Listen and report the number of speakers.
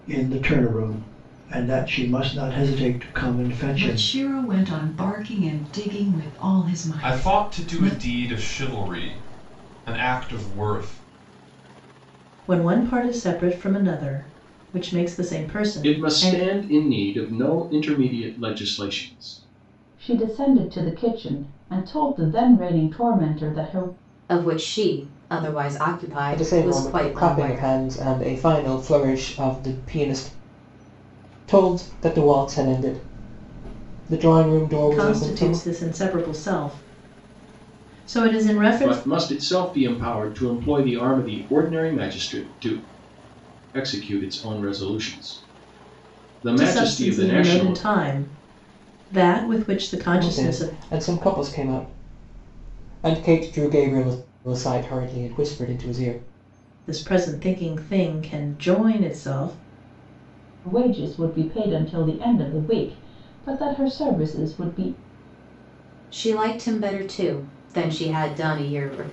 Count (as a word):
eight